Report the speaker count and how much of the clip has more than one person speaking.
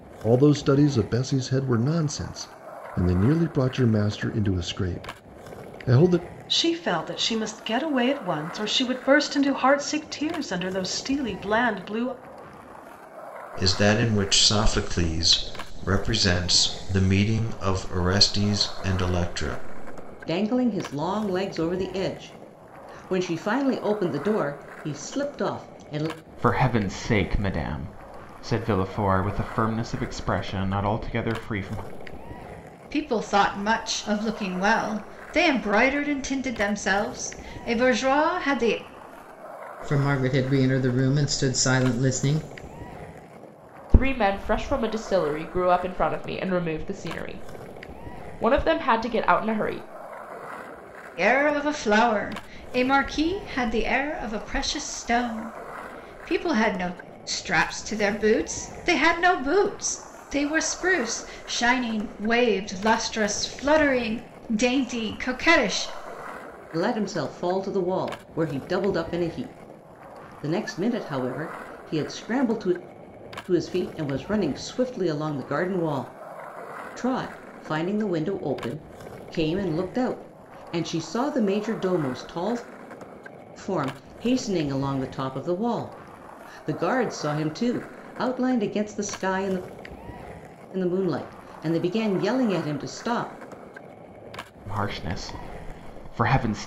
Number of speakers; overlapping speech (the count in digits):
8, no overlap